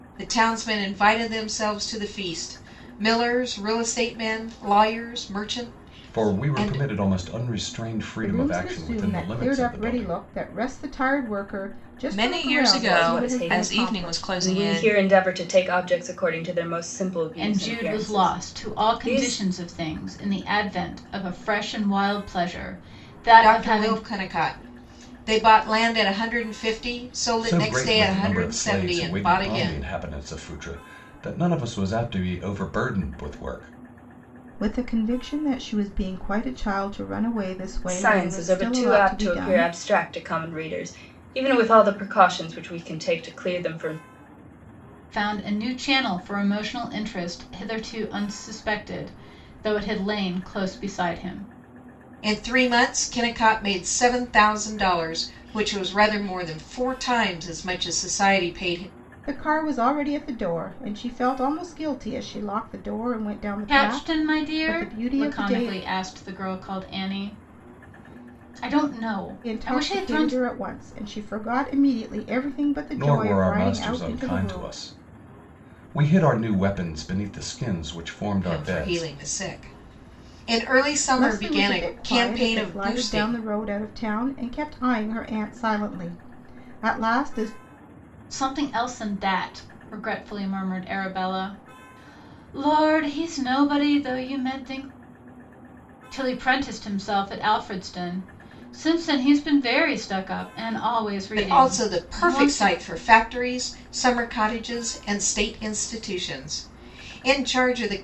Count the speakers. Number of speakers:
six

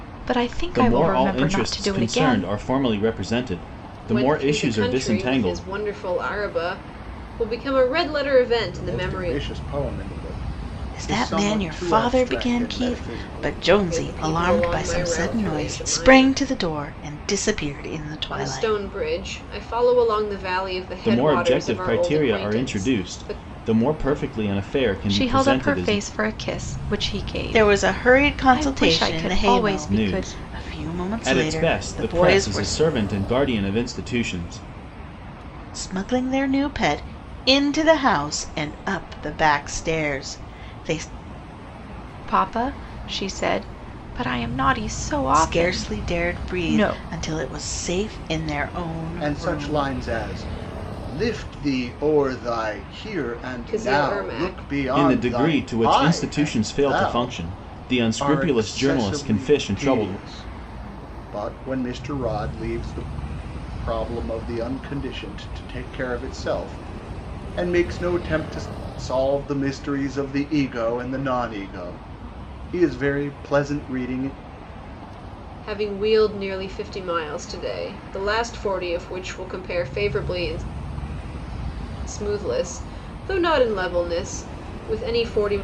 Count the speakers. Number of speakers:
five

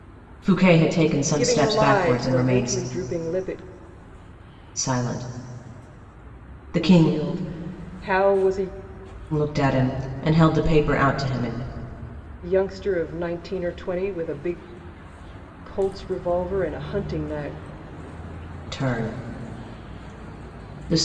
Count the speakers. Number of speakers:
two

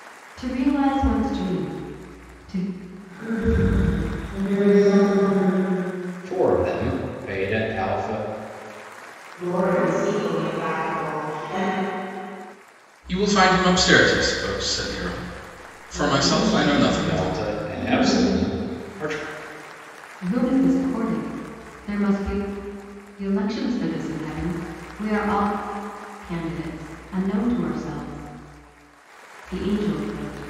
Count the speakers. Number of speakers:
five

